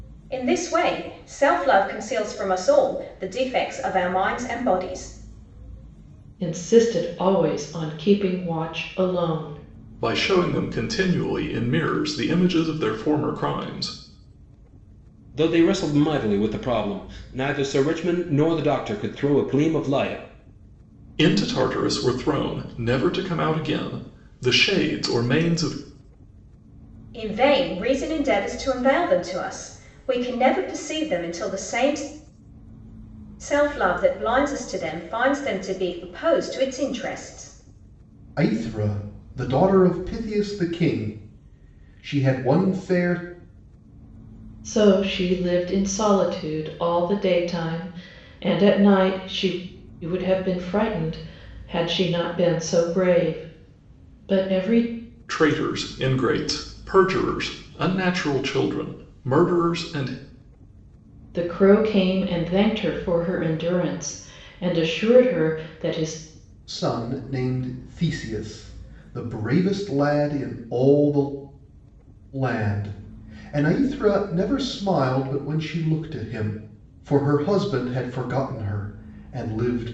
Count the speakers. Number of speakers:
4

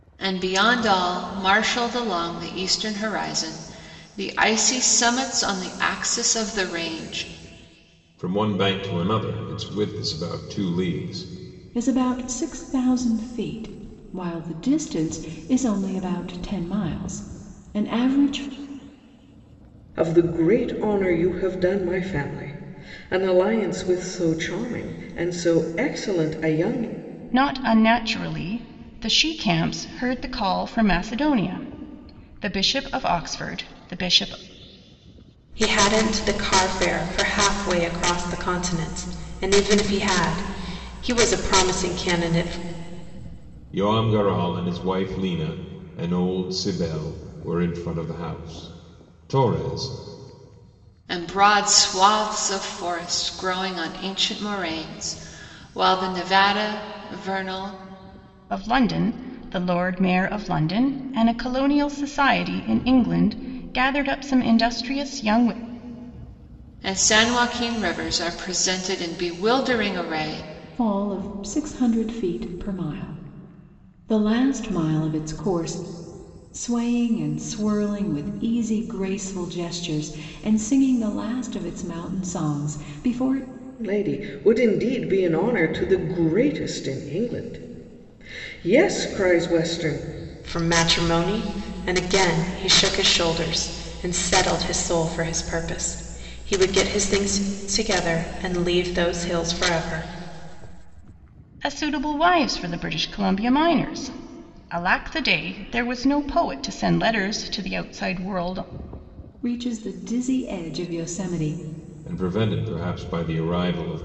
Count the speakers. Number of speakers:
6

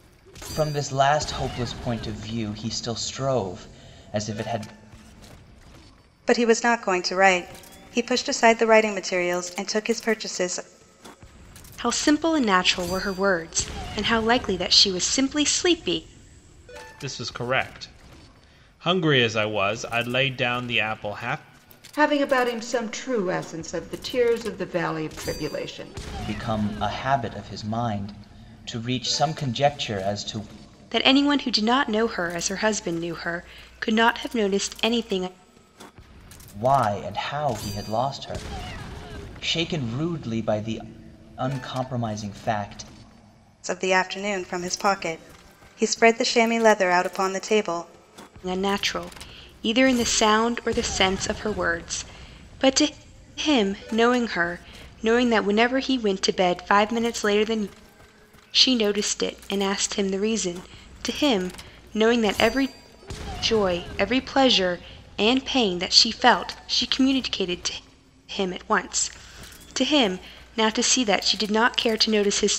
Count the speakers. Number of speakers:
5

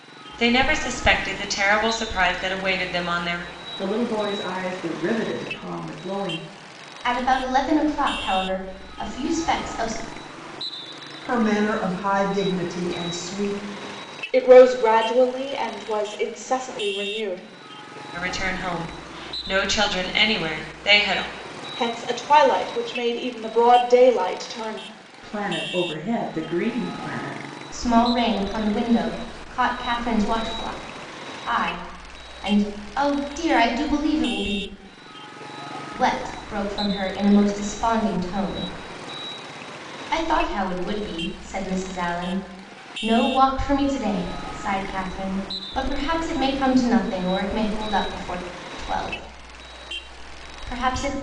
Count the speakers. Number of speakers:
5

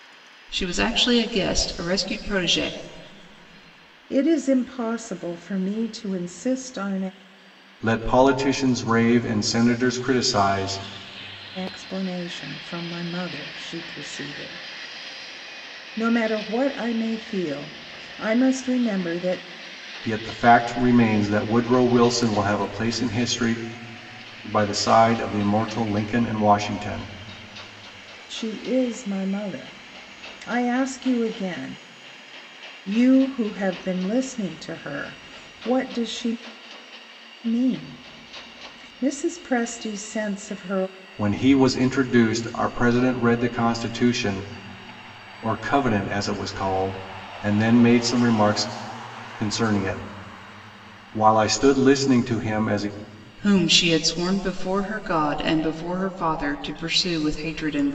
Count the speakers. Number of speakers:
3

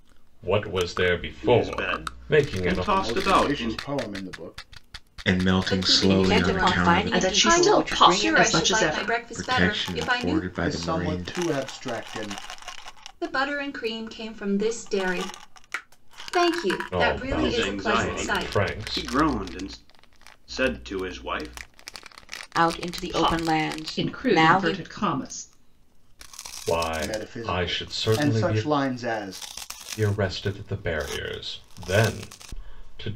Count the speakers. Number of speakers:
7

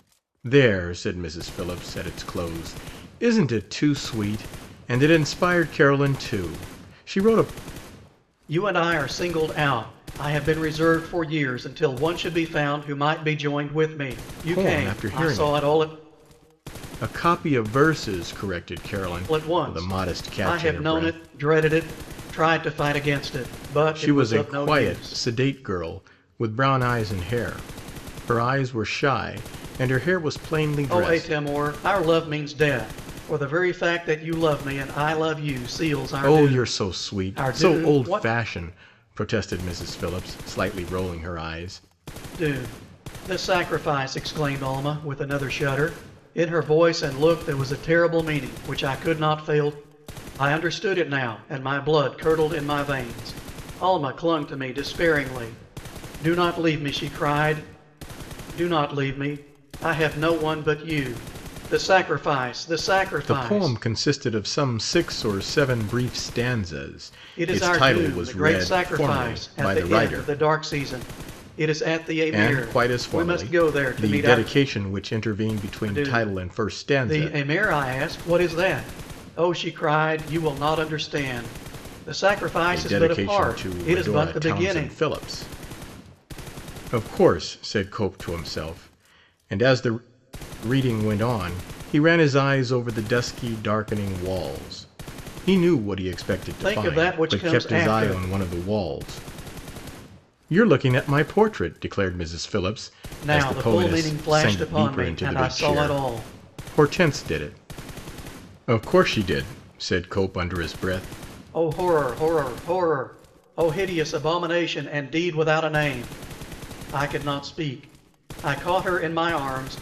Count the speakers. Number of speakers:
2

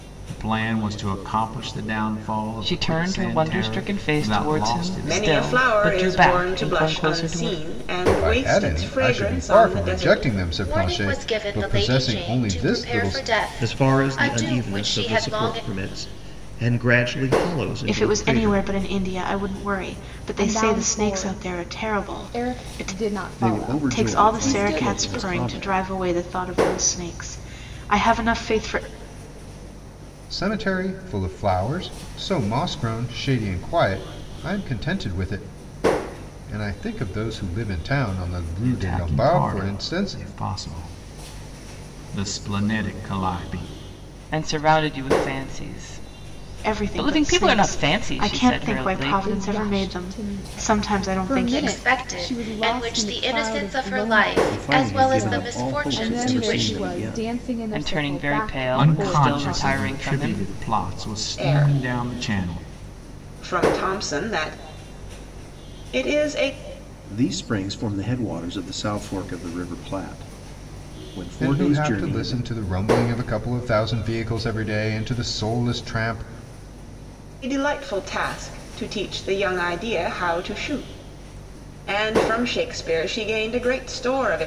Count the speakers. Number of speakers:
9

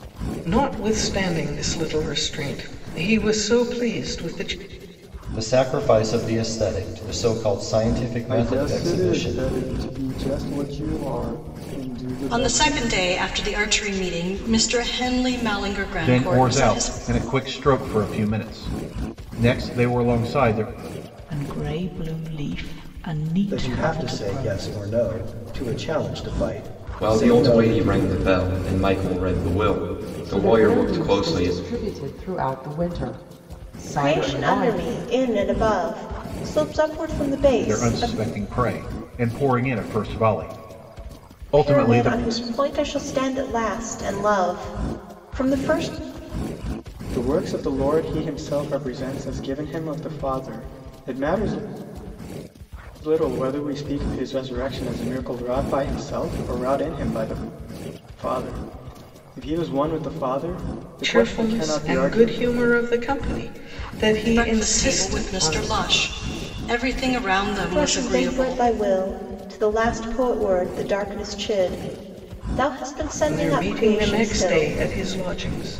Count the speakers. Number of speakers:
10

